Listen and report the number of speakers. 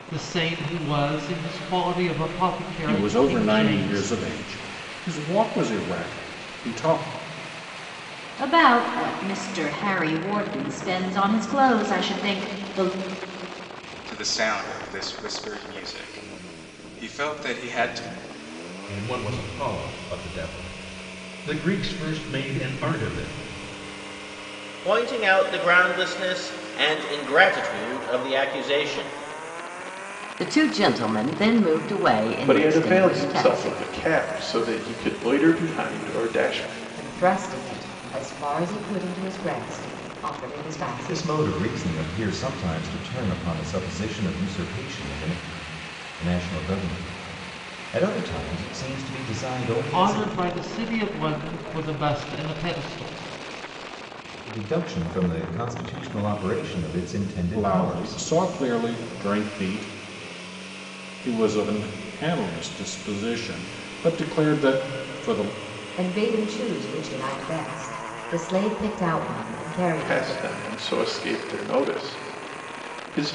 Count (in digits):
10